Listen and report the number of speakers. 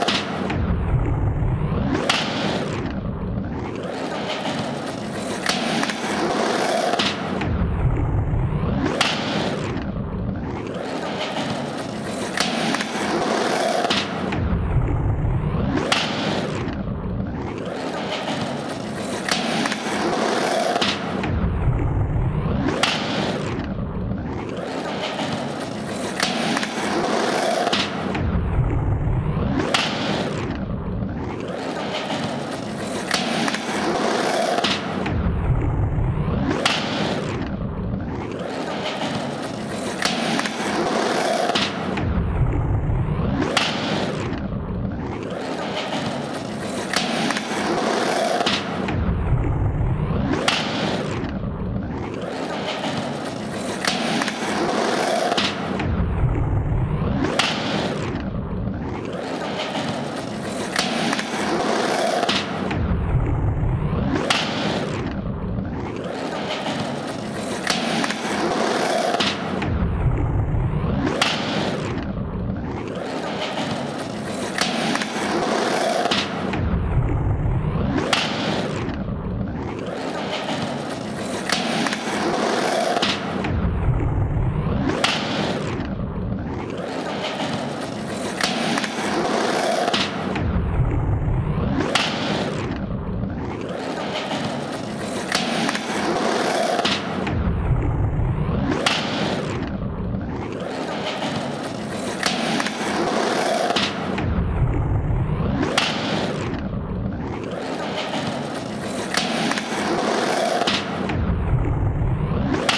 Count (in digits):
0